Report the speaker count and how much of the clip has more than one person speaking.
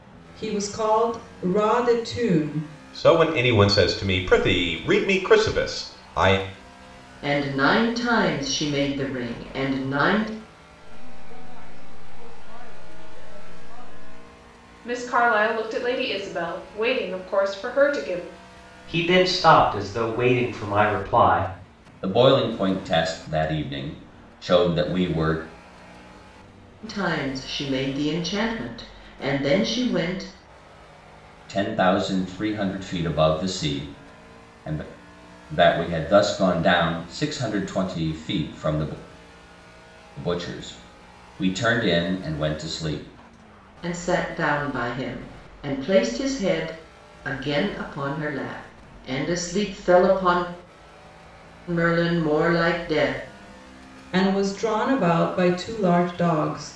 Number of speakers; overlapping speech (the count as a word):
seven, no overlap